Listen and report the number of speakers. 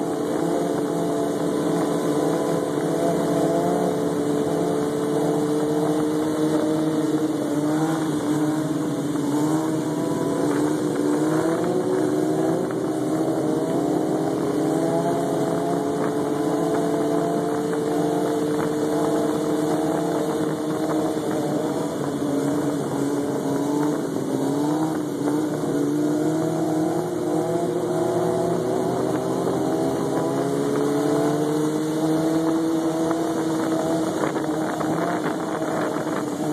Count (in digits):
0